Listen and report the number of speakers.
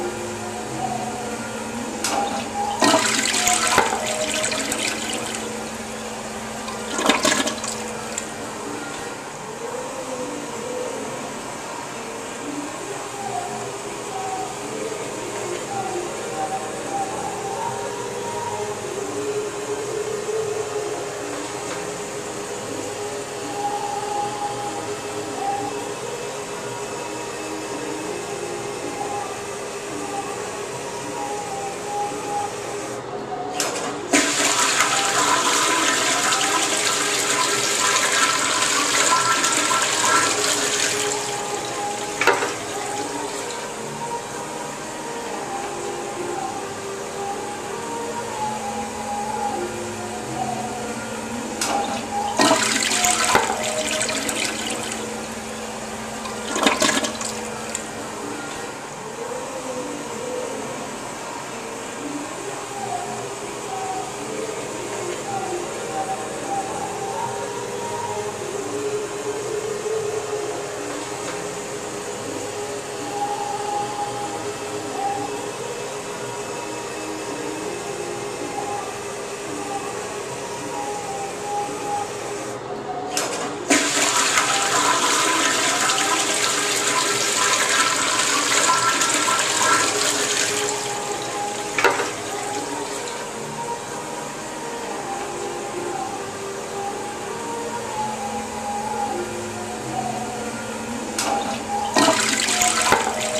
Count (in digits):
0